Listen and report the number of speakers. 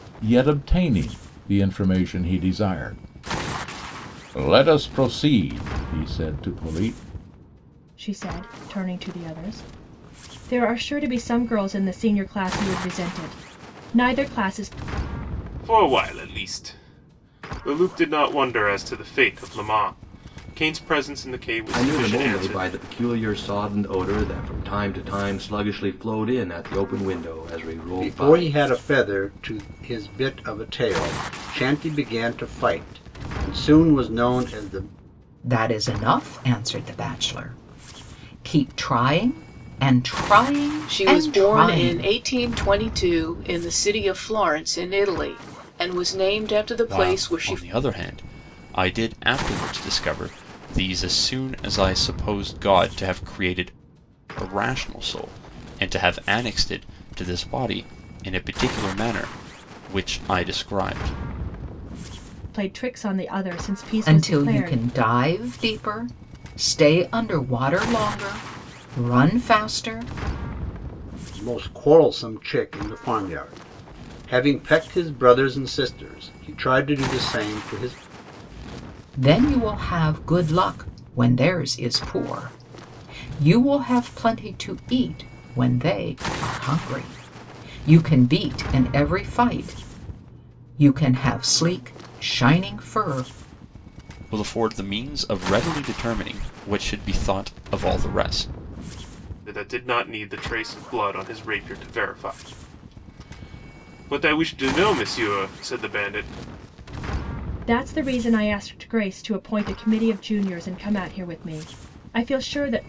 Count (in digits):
8